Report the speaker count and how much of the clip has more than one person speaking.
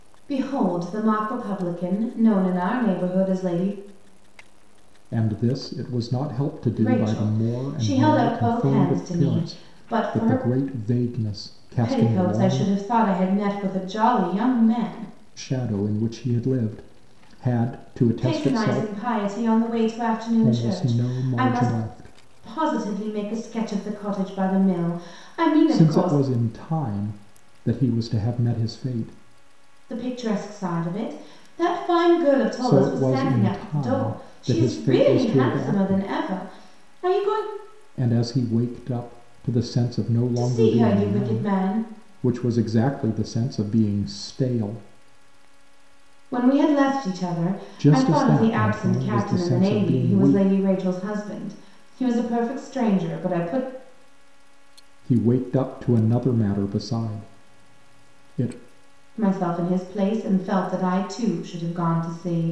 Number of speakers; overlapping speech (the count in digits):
2, about 24%